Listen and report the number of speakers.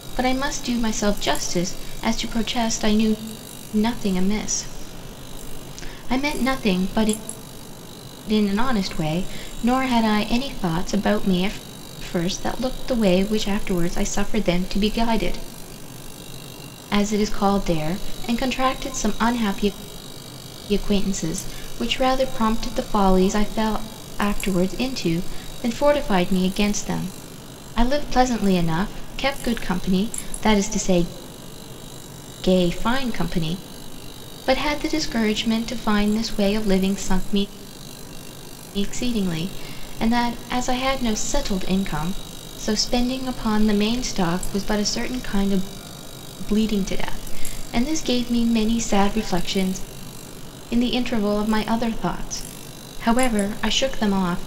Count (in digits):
1